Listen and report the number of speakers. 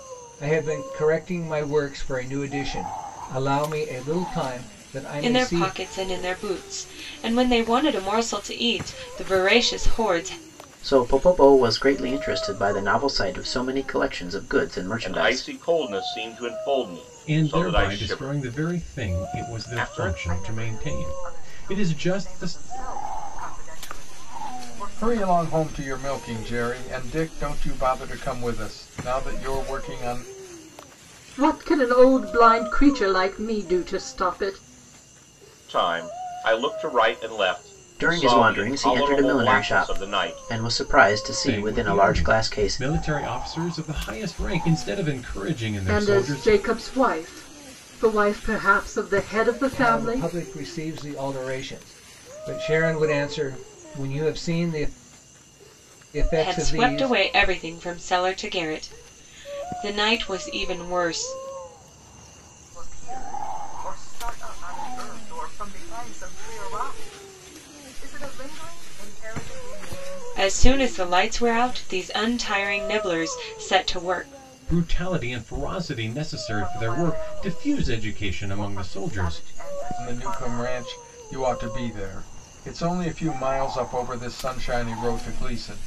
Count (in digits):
8